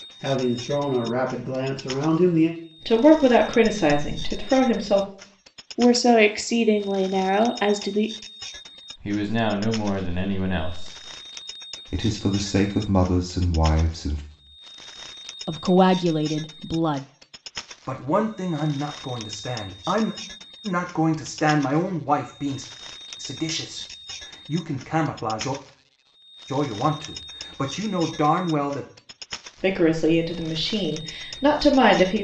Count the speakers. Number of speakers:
7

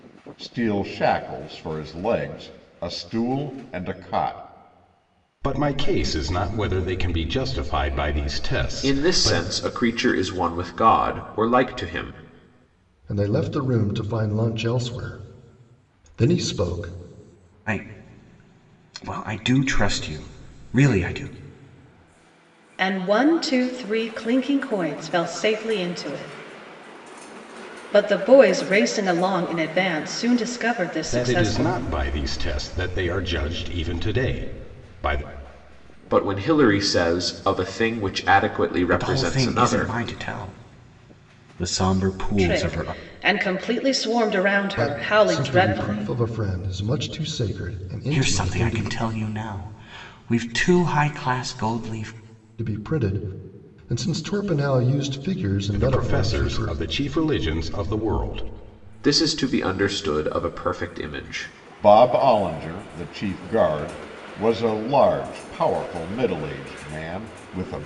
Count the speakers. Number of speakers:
6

